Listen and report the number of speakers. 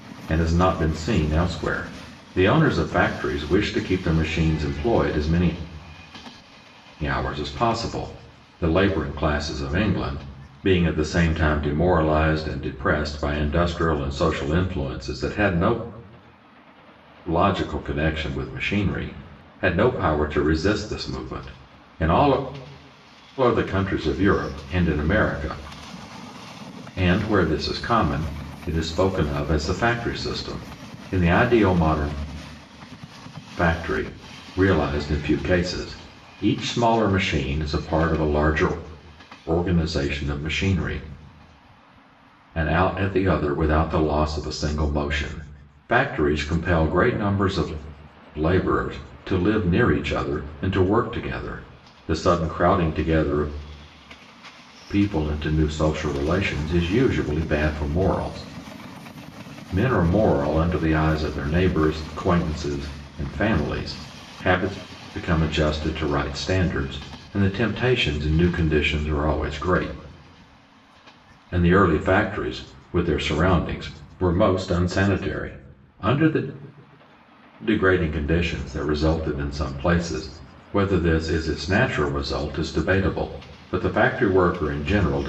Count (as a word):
one